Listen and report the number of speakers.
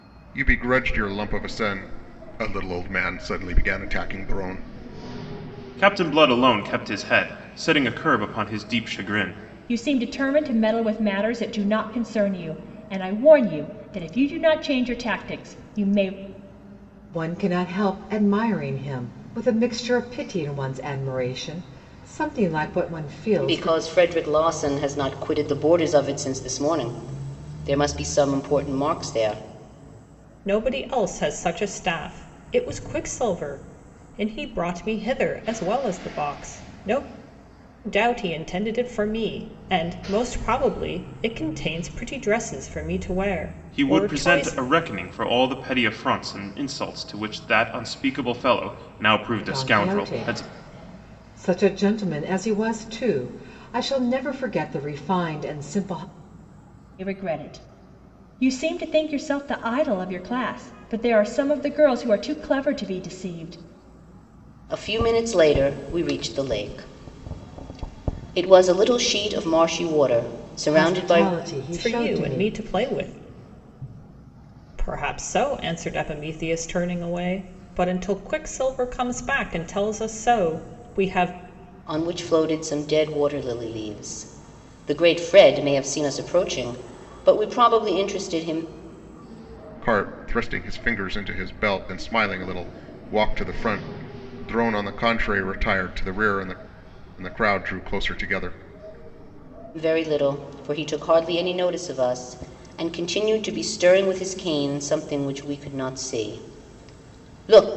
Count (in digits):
6